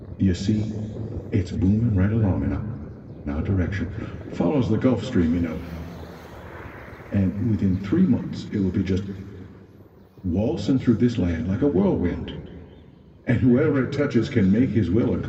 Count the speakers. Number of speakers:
1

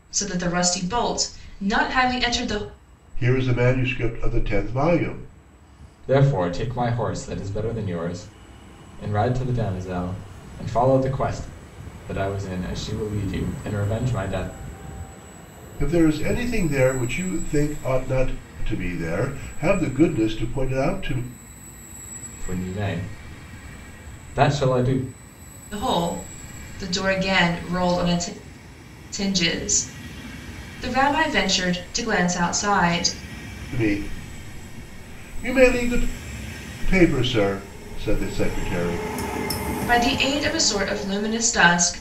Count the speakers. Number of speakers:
3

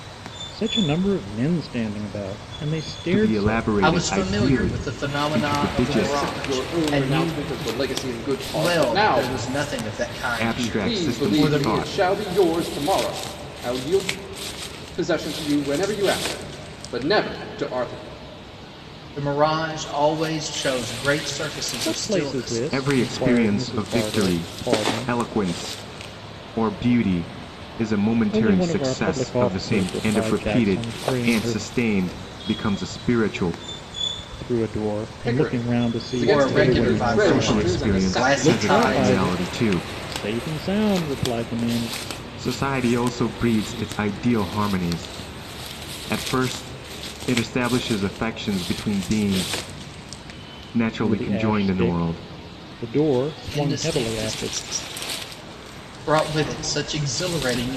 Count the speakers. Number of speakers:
4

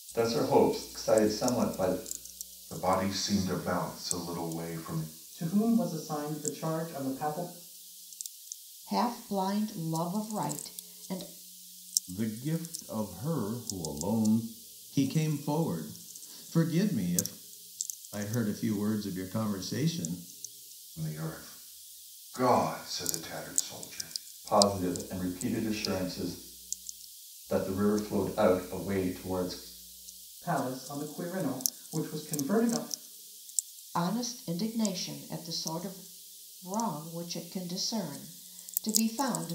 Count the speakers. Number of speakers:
6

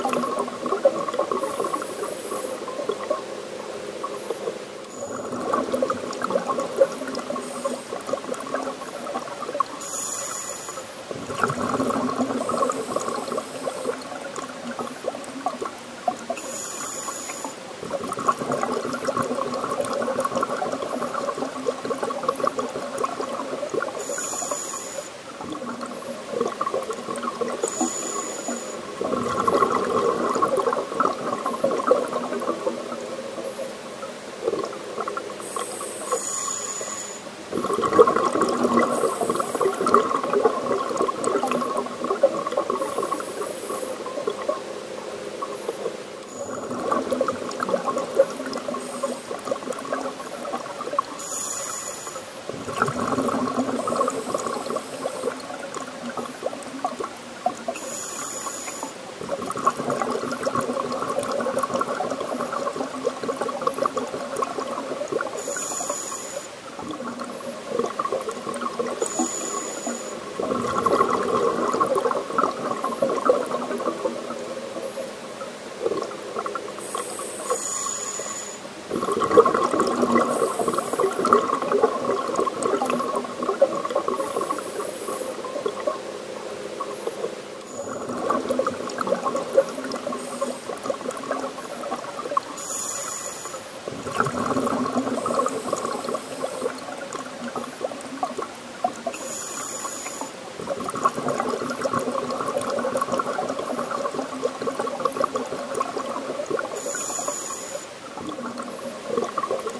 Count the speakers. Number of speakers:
0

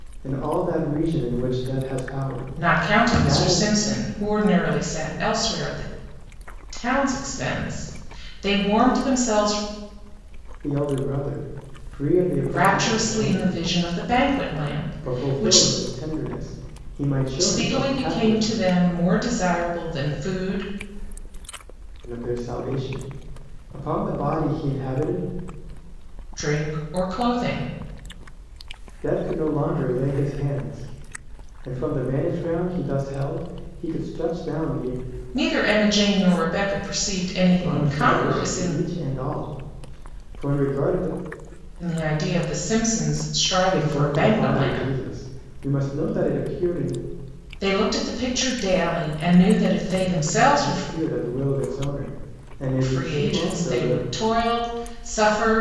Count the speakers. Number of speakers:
2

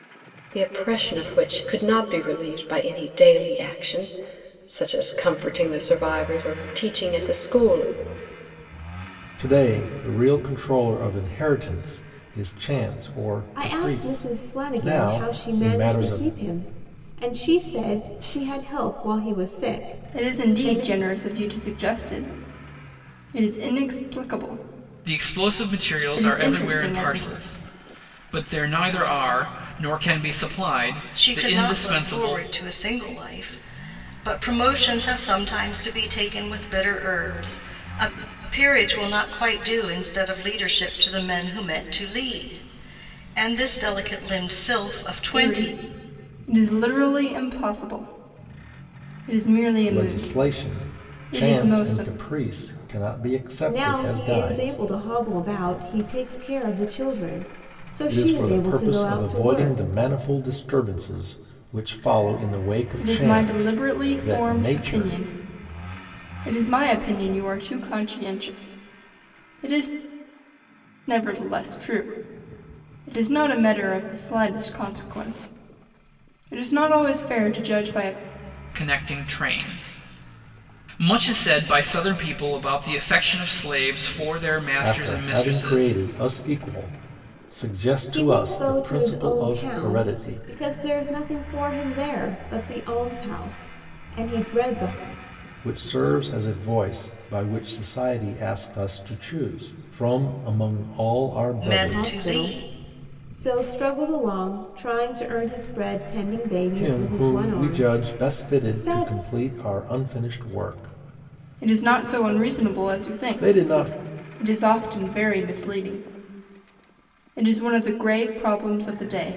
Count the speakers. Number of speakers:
6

